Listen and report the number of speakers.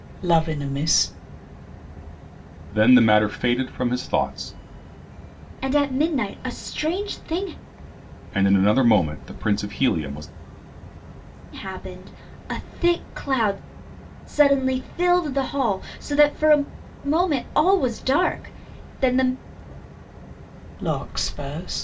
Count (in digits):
3